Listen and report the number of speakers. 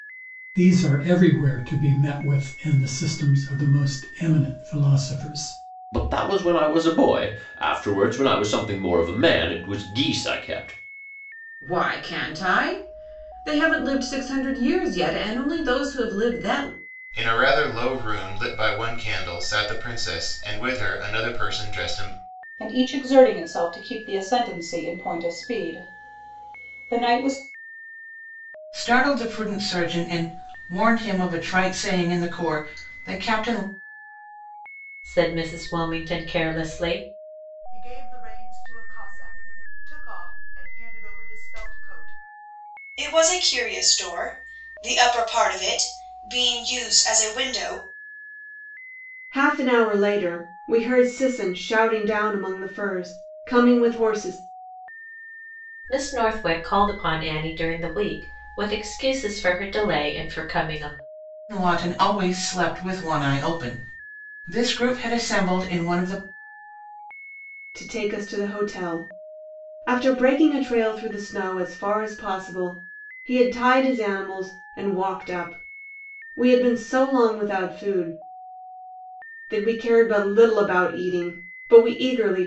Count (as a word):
ten